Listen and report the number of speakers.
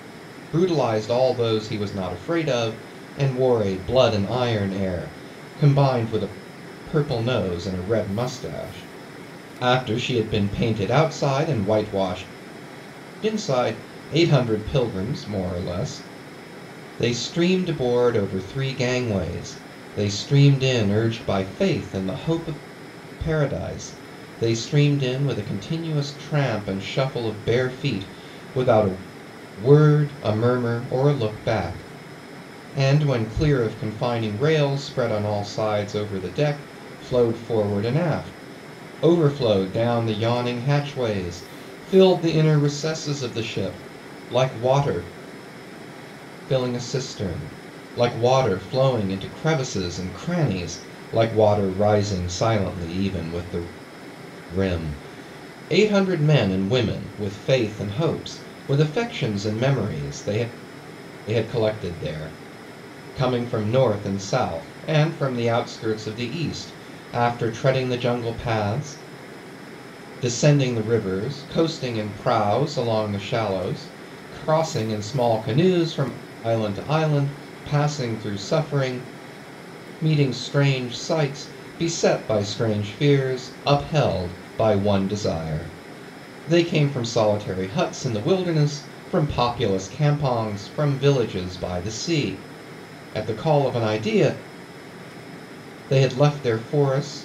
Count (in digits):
1